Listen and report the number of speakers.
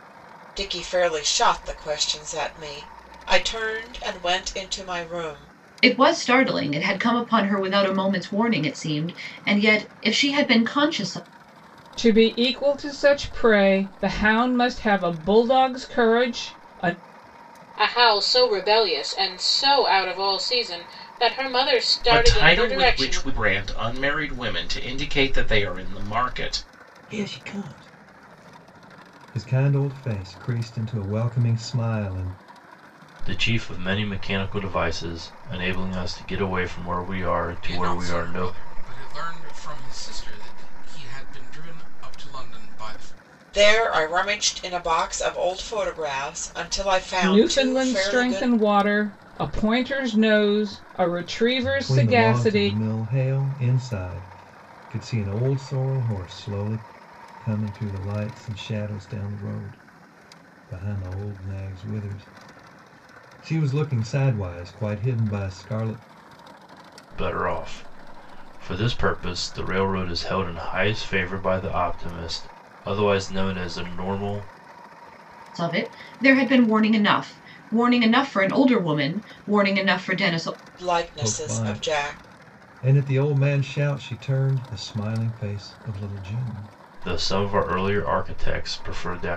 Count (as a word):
eight